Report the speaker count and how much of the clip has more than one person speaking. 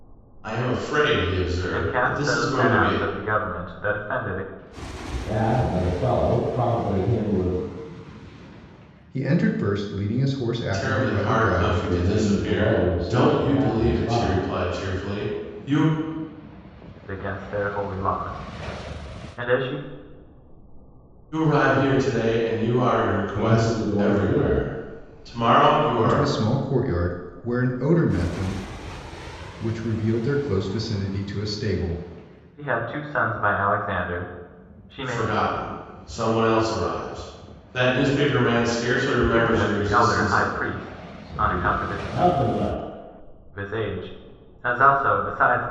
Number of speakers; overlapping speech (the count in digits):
4, about 19%